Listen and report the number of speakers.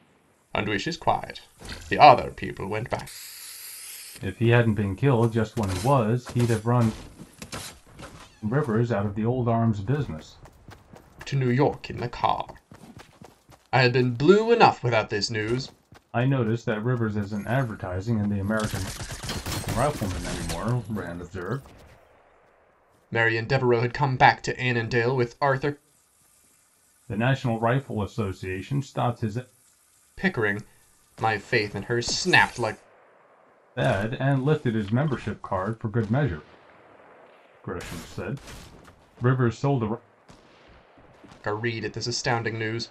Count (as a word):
two